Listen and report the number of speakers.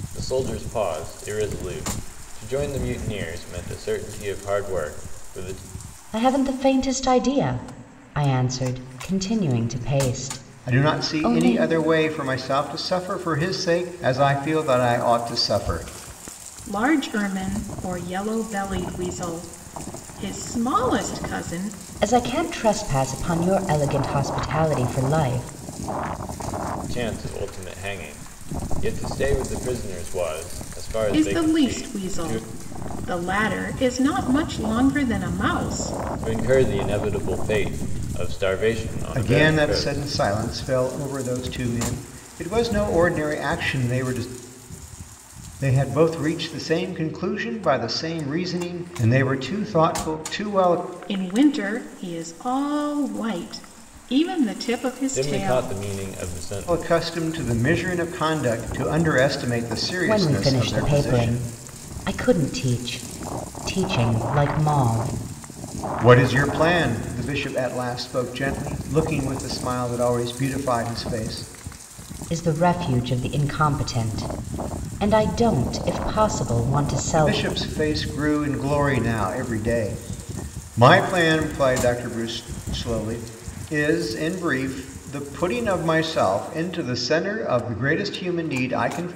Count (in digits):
4